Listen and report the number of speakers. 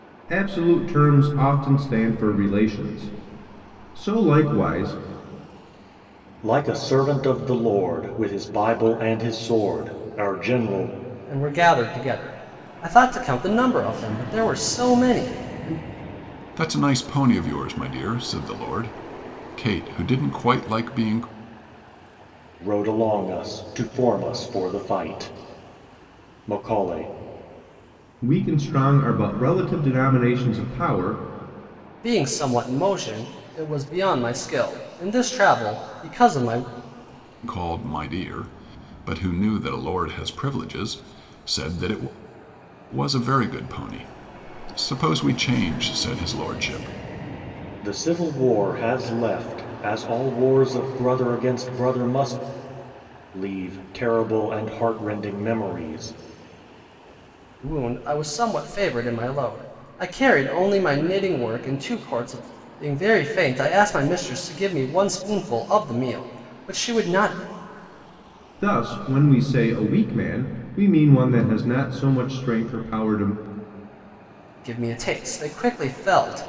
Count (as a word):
four